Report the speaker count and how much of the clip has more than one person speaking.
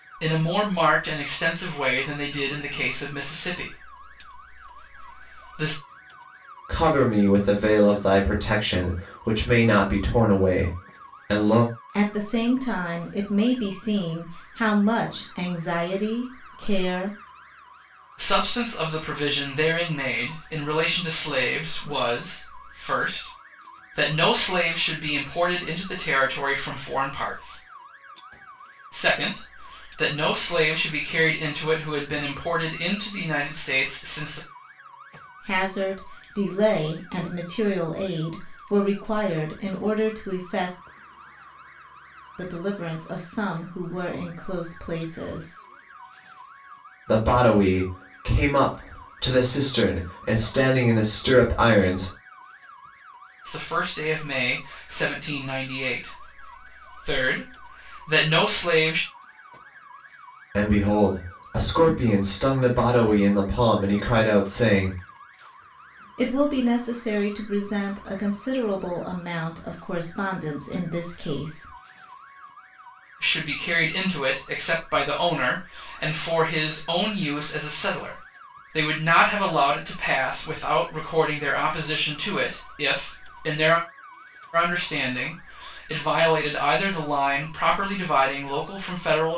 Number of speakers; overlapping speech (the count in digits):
3, no overlap